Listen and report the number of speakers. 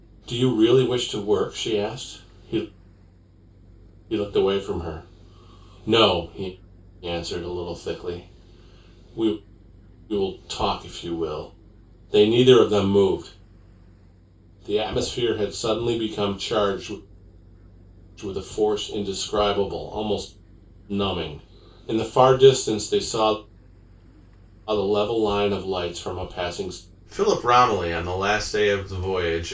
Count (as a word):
one